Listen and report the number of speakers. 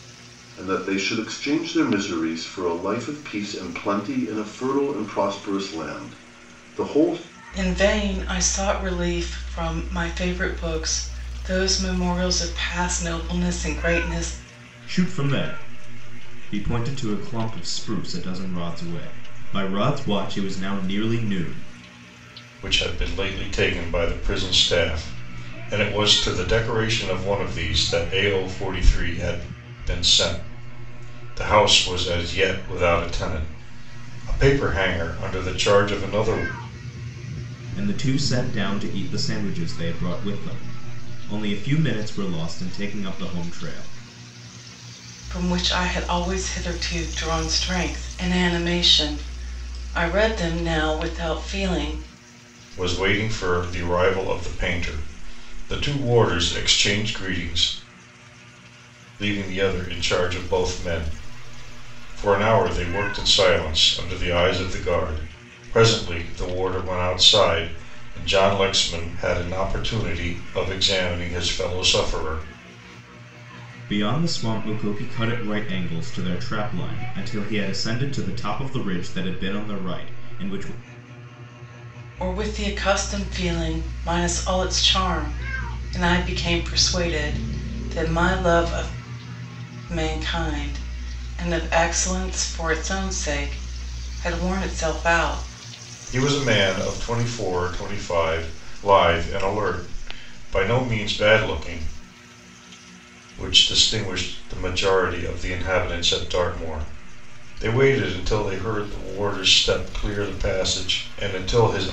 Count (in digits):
4